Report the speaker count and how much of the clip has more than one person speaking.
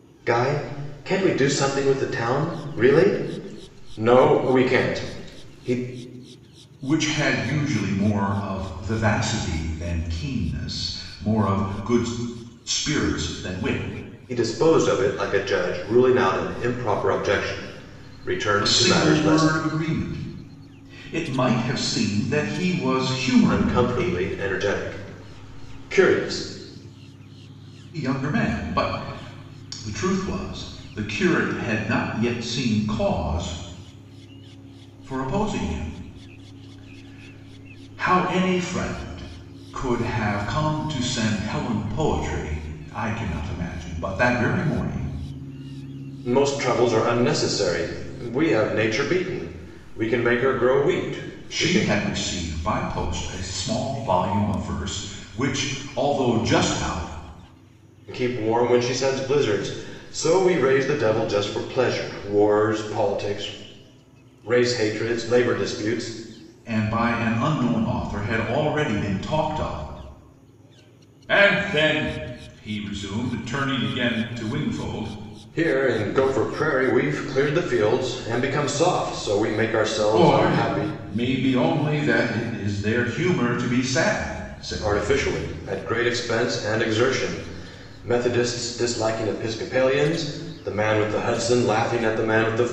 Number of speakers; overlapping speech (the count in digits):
2, about 4%